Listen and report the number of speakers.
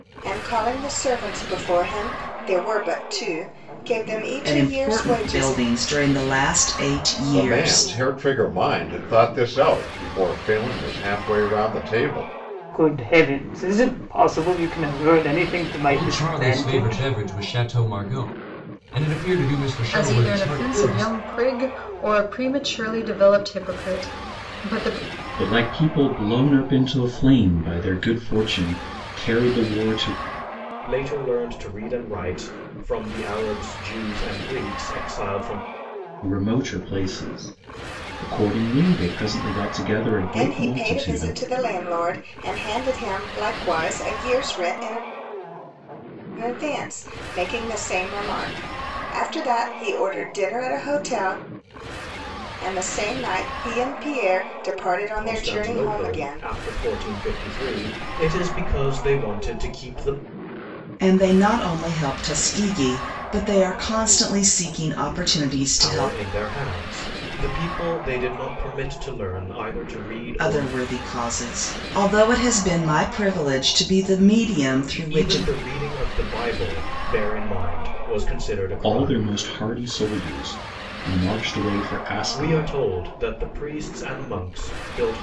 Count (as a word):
eight